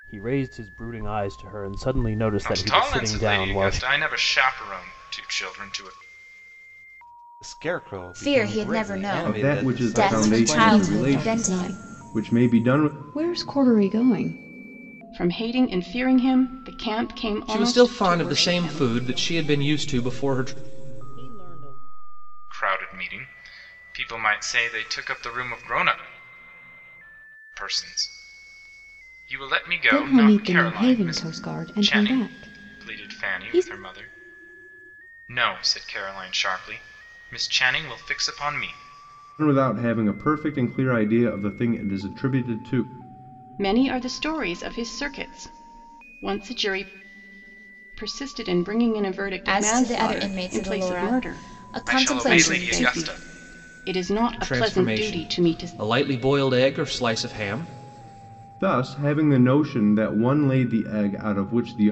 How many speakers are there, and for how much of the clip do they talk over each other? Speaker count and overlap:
9, about 28%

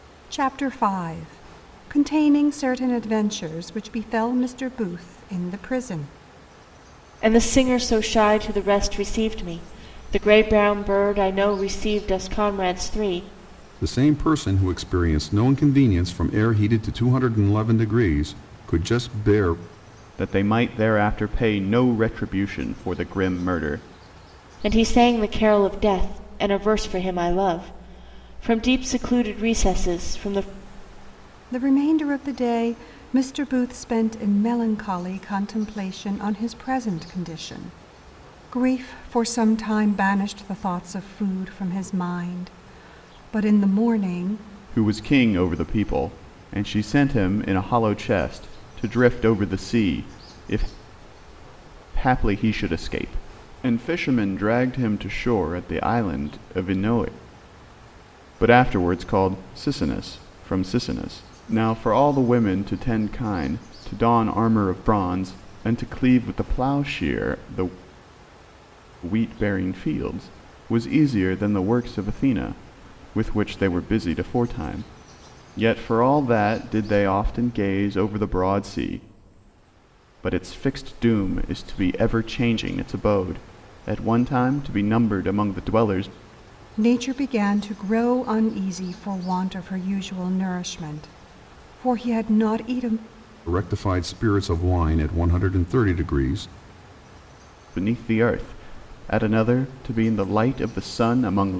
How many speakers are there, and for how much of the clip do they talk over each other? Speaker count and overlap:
4, no overlap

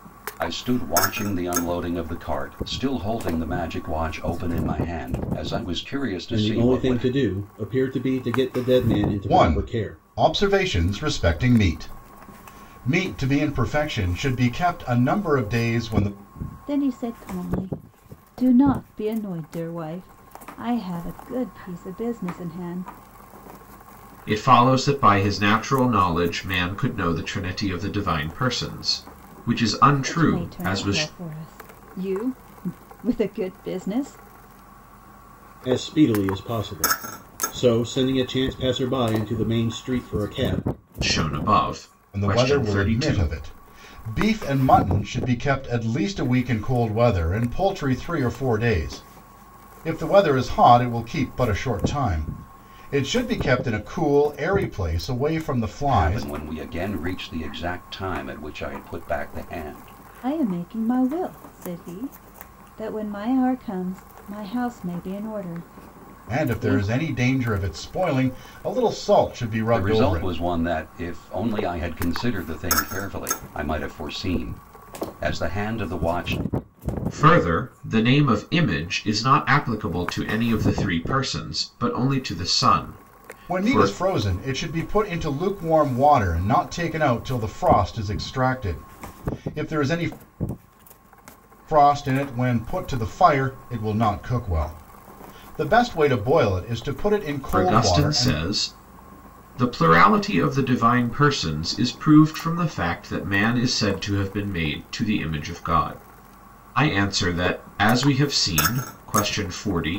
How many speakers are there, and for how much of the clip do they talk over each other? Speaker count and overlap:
5, about 6%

